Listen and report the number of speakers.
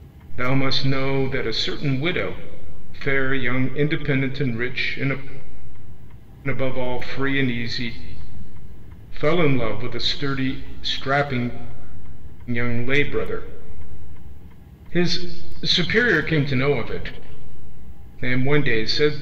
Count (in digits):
1